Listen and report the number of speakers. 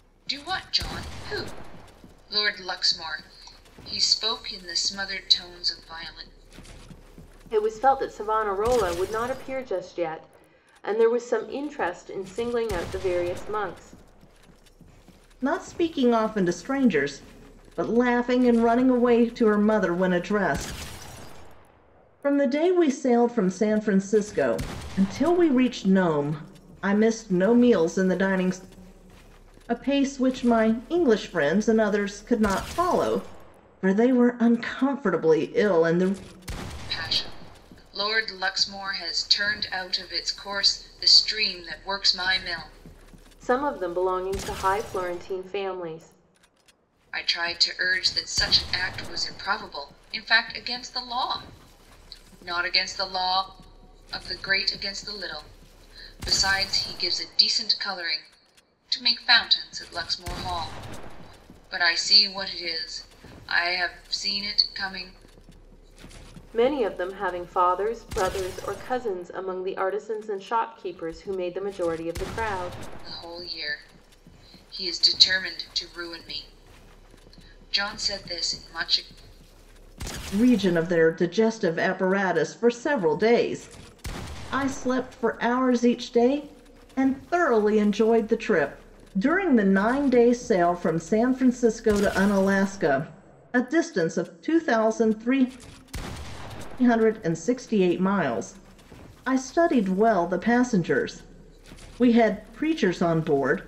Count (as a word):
three